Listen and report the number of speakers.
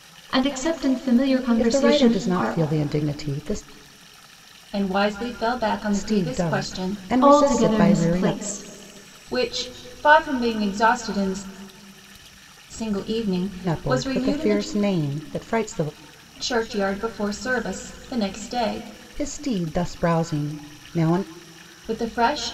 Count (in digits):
3